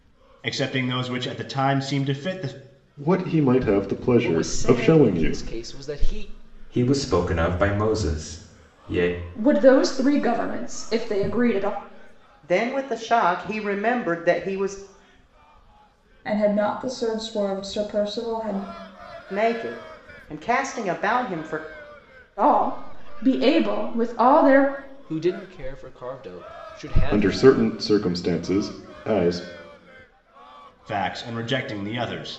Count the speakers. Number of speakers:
seven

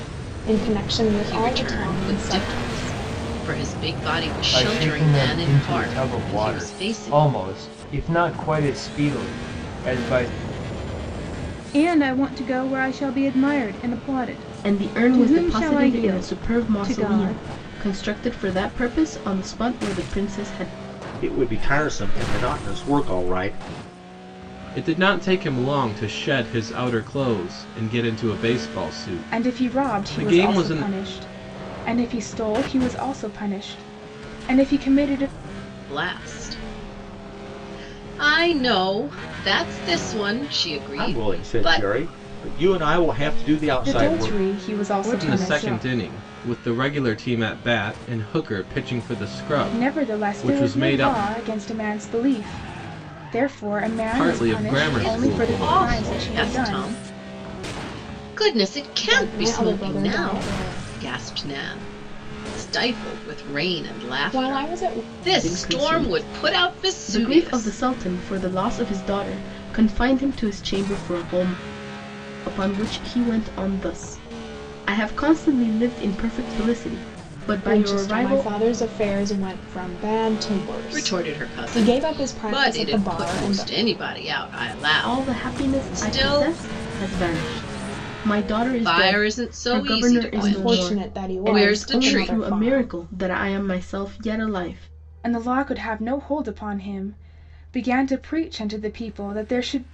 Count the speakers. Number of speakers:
eight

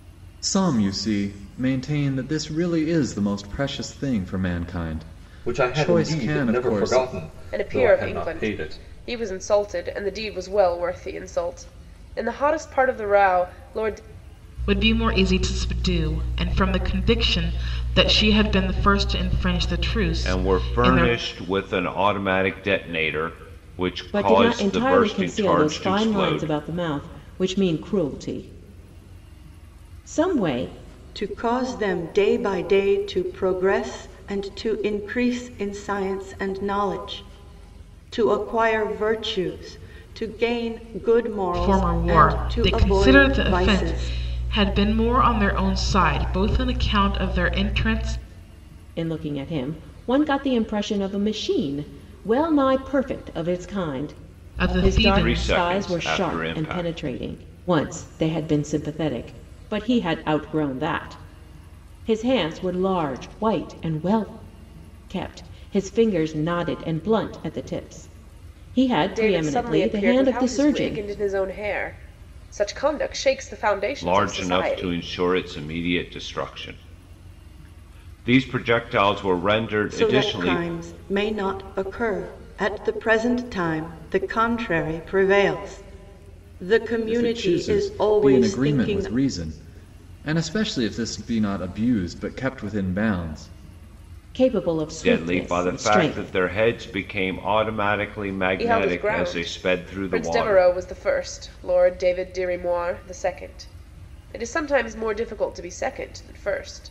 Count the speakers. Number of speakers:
seven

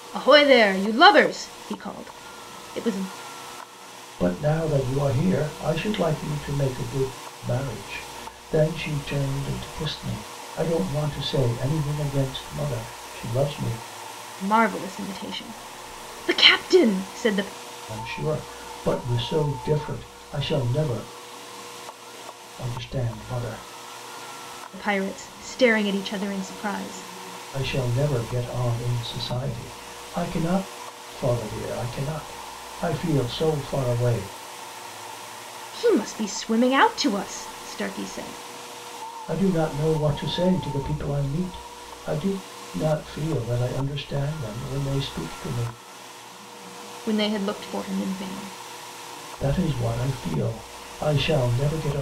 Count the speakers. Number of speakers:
two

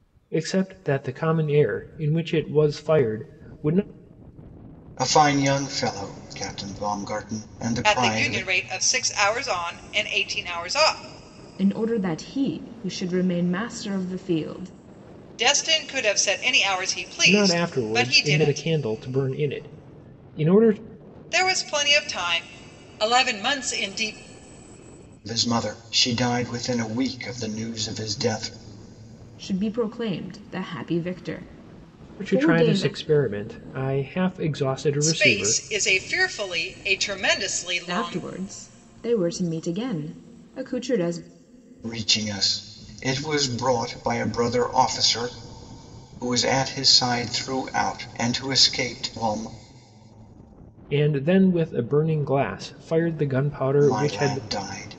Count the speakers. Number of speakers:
four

